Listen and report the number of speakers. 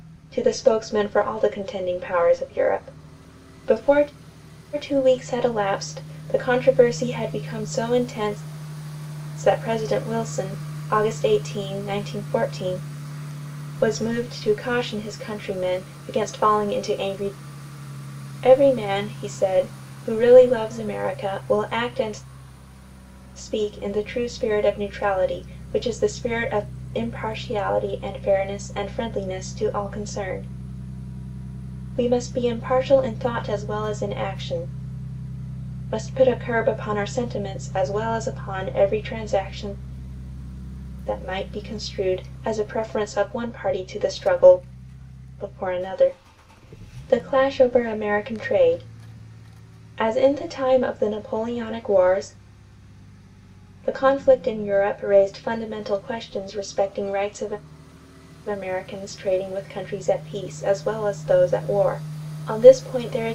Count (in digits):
1